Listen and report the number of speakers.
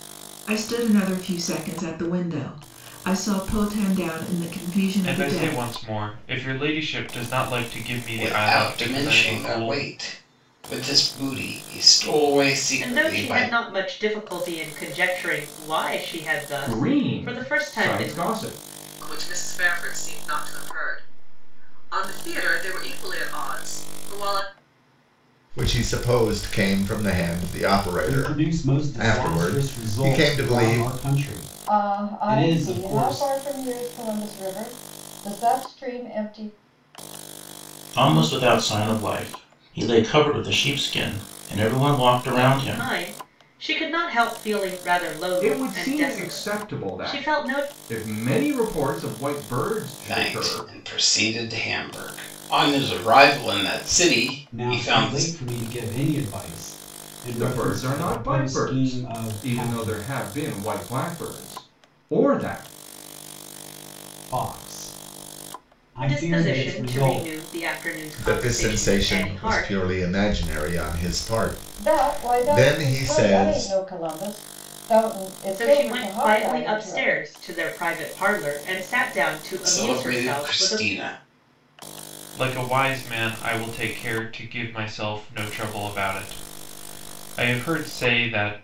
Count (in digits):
10